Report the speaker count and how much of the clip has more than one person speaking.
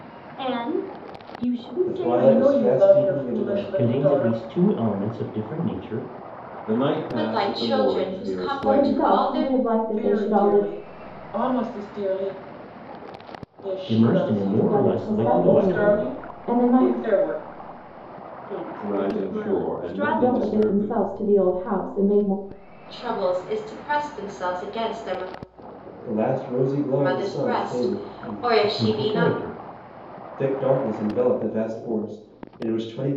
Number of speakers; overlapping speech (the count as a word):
seven, about 41%